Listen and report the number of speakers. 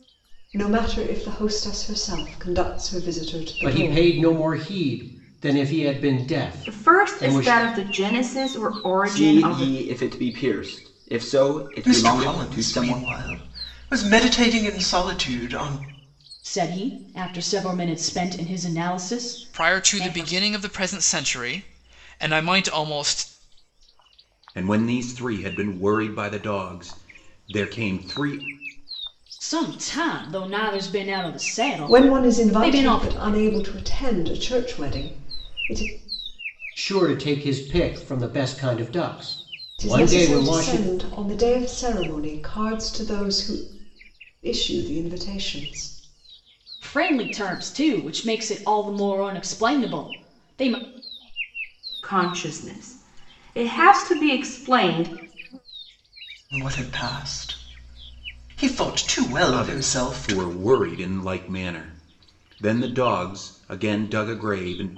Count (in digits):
8